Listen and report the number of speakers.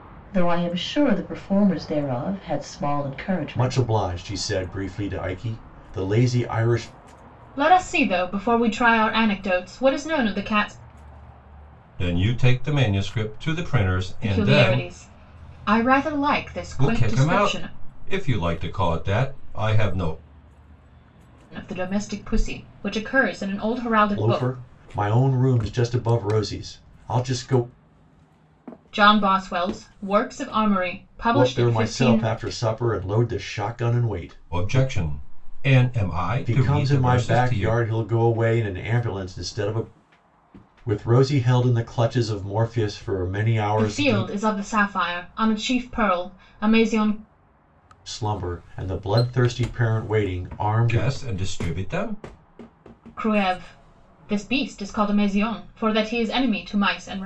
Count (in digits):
4